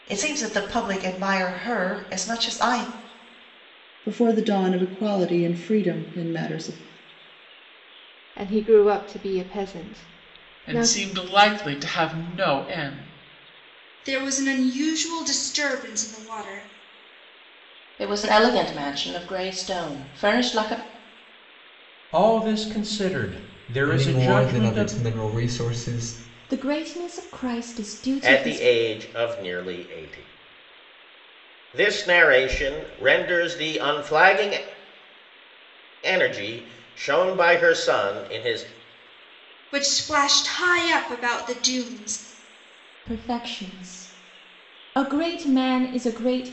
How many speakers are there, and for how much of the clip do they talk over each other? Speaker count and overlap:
10, about 4%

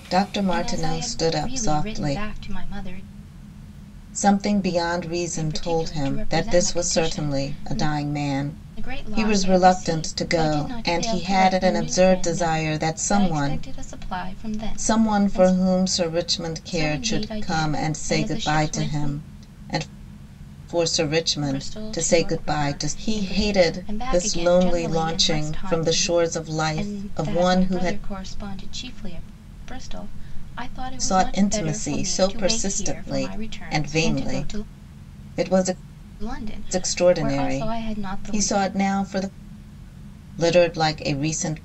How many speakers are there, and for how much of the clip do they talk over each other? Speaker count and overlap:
2, about 56%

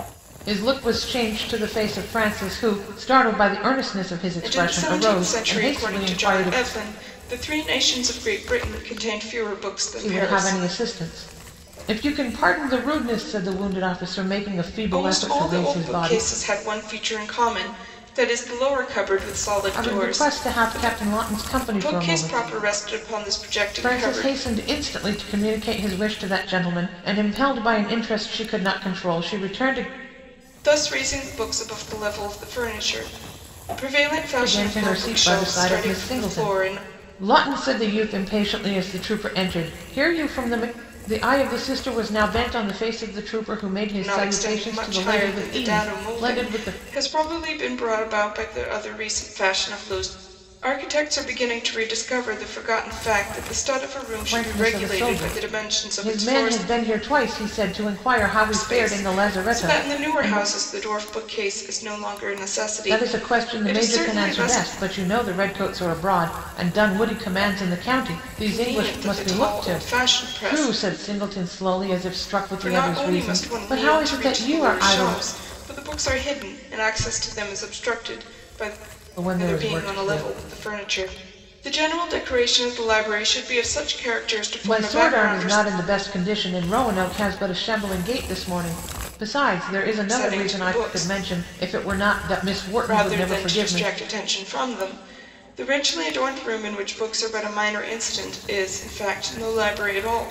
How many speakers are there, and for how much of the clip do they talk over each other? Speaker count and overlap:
2, about 27%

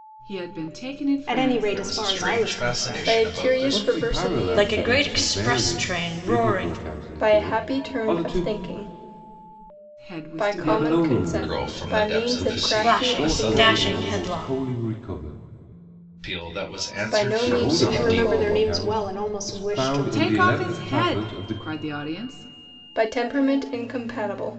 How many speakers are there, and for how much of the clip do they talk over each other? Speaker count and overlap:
6, about 63%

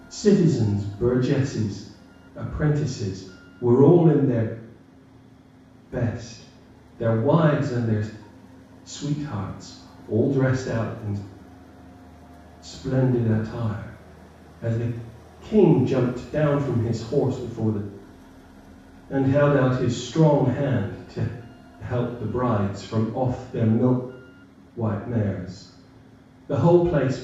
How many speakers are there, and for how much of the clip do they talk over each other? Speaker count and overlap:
1, no overlap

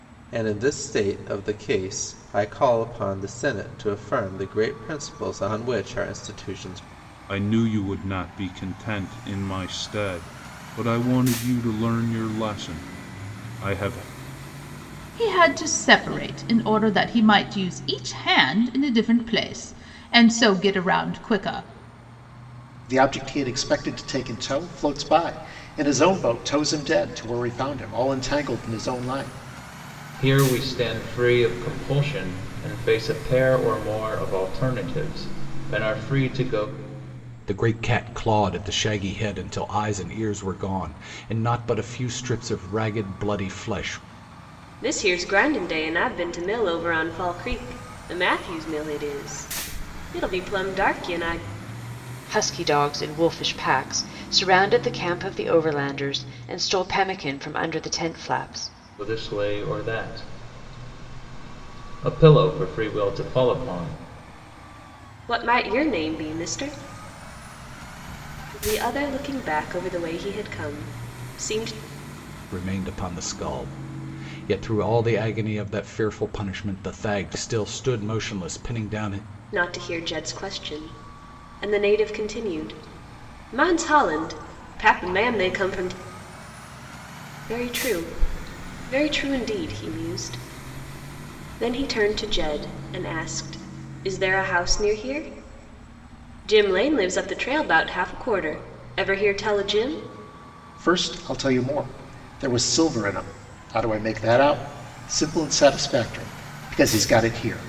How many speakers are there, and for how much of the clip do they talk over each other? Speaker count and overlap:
8, no overlap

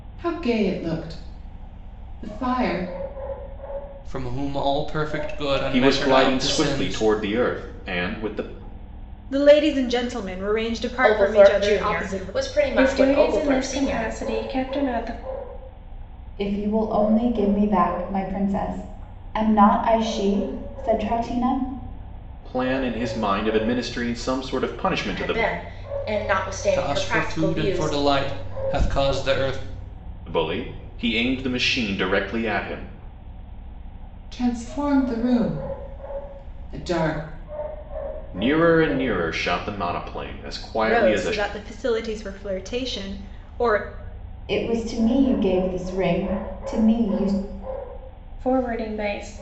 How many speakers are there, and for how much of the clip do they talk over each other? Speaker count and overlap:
7, about 13%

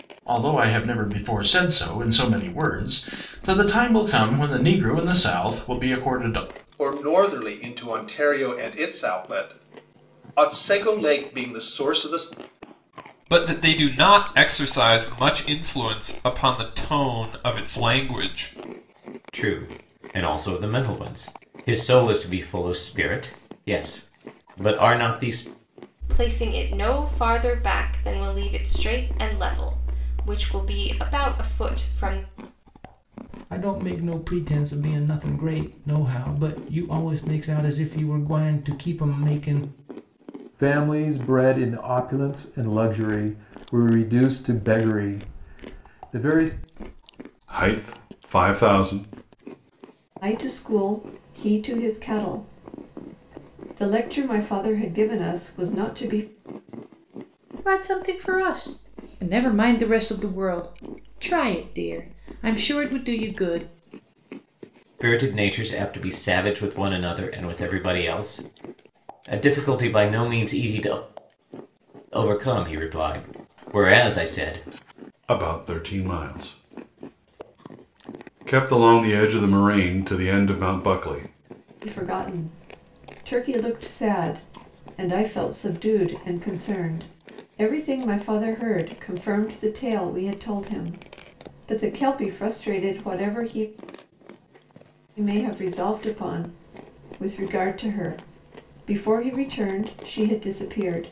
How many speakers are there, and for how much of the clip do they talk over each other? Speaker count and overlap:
10, no overlap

